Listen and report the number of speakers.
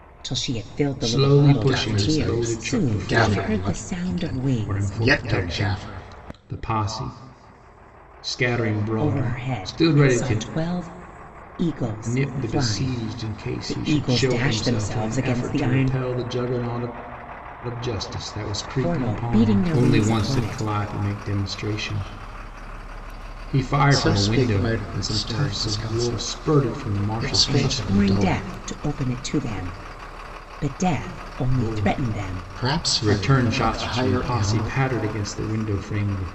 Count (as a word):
three